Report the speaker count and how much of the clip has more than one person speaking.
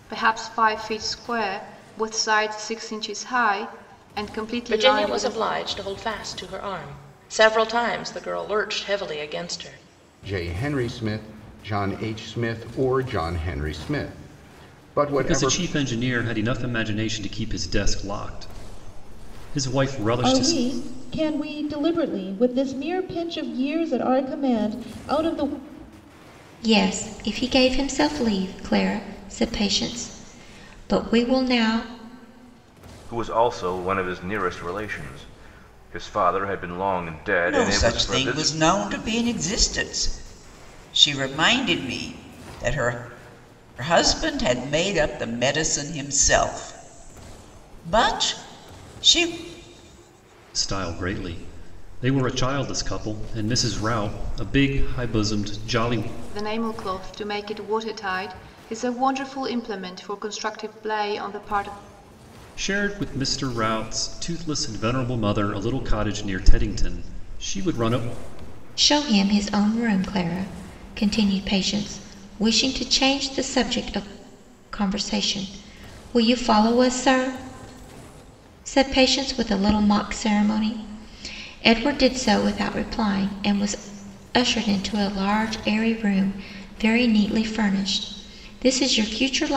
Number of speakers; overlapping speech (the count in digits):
8, about 3%